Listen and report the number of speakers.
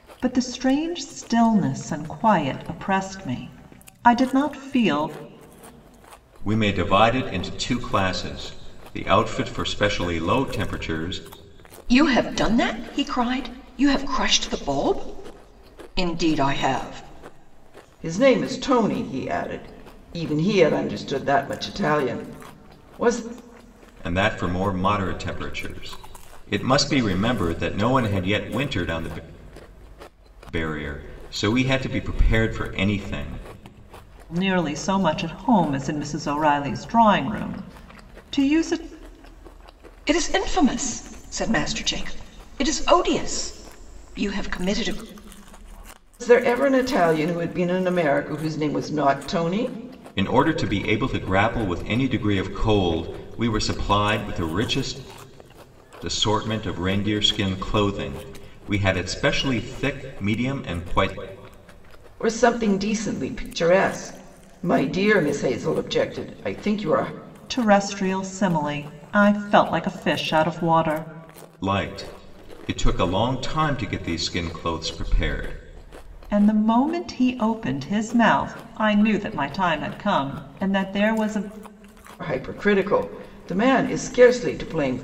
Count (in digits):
4